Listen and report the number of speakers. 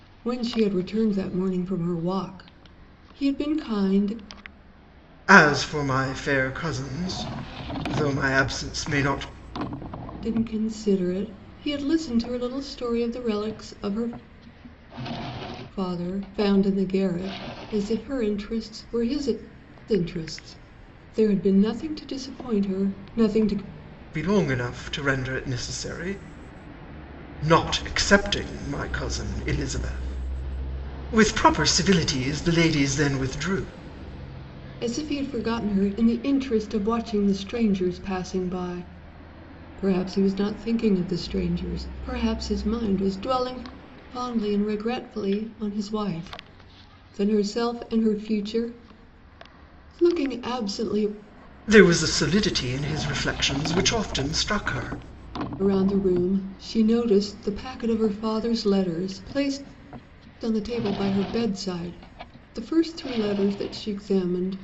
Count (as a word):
two